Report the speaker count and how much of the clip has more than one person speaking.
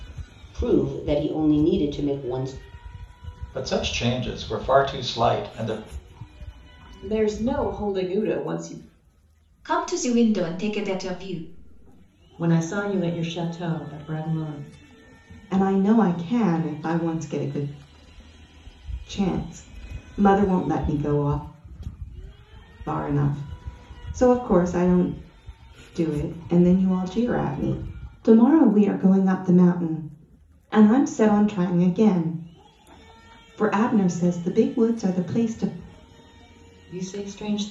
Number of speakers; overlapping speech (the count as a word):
six, no overlap